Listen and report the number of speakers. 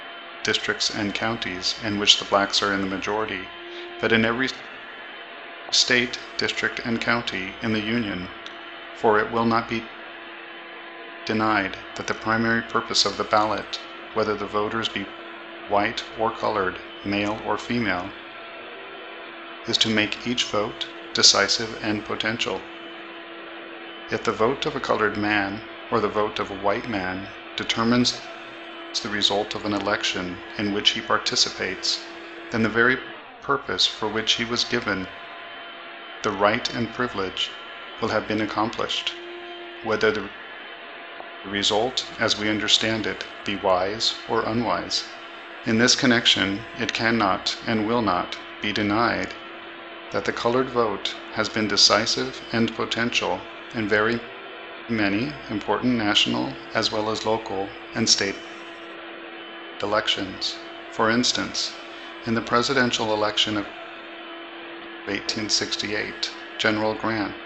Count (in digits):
1